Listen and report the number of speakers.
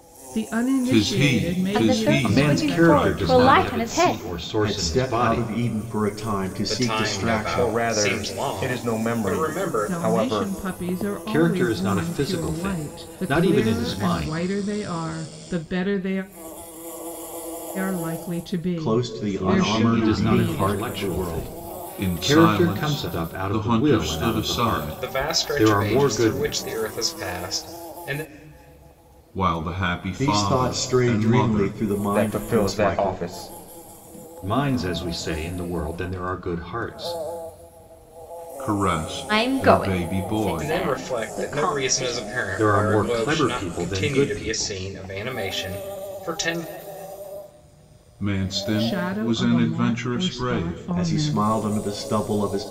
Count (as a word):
seven